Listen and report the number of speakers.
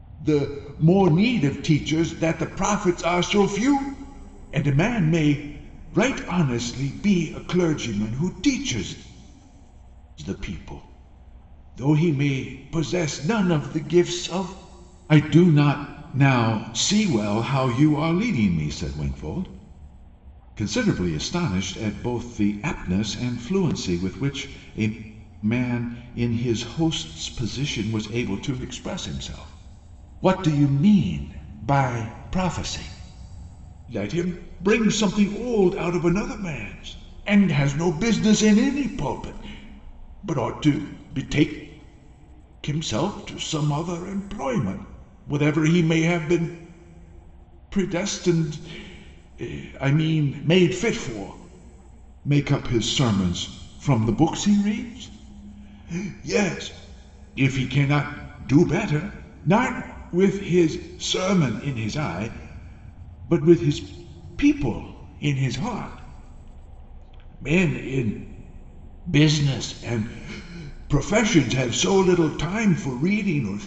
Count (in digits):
1